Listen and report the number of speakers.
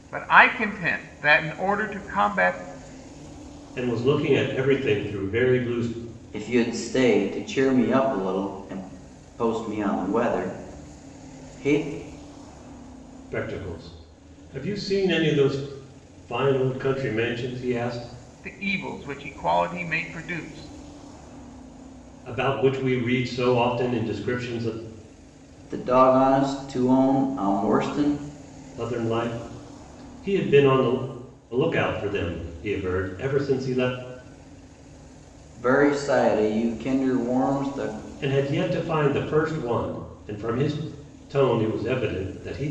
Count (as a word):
three